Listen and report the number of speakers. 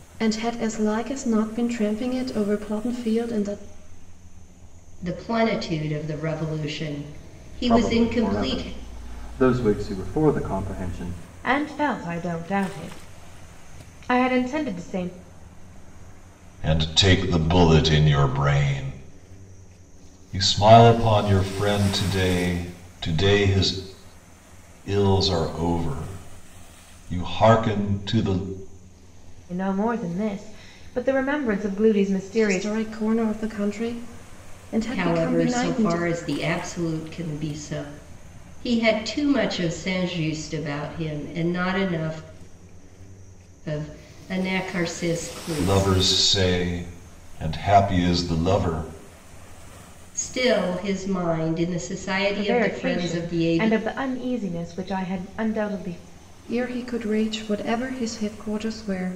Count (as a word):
five